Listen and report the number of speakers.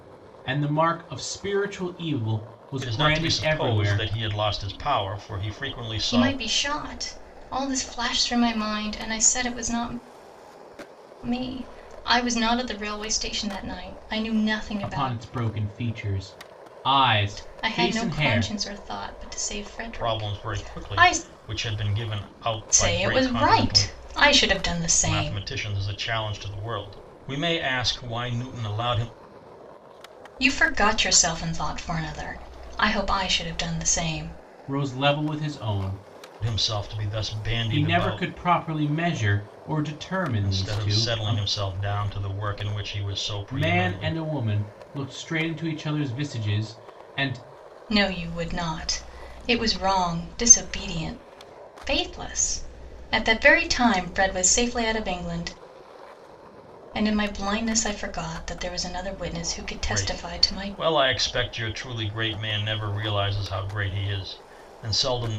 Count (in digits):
3